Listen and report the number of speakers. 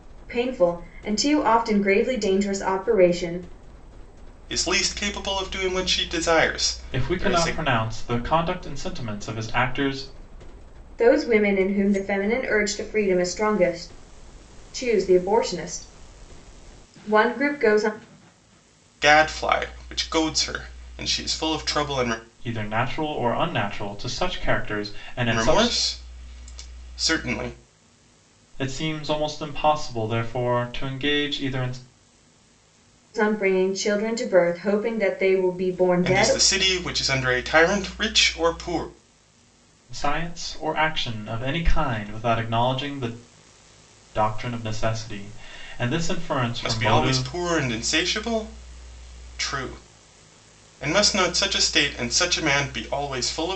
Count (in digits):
3